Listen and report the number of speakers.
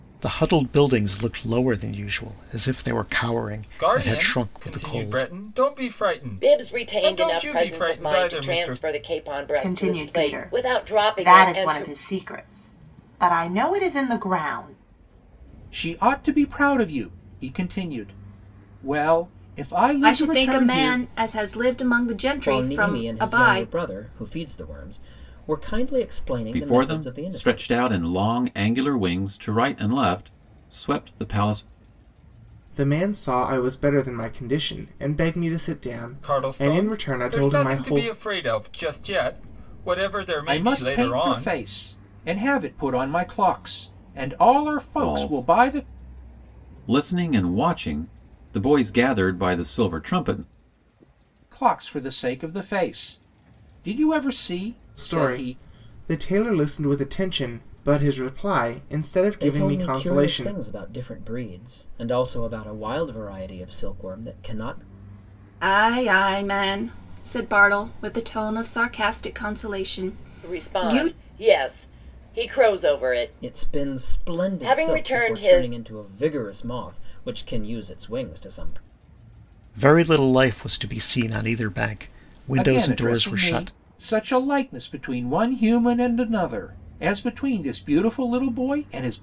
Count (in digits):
9